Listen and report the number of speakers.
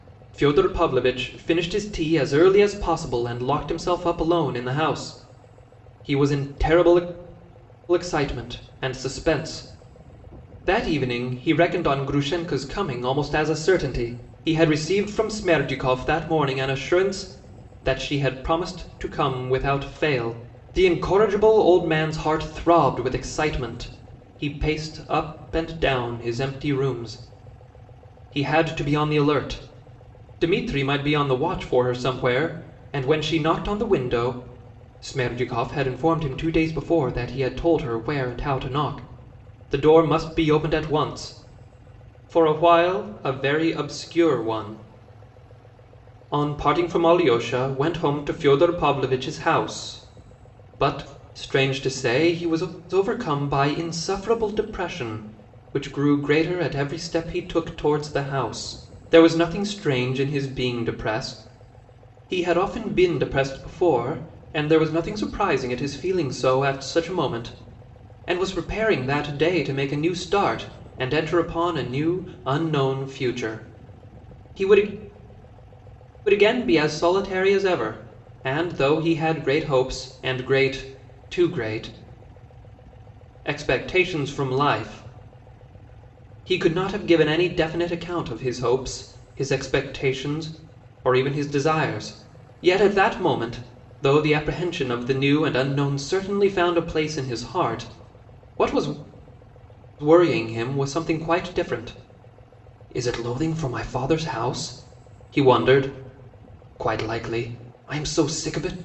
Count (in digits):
1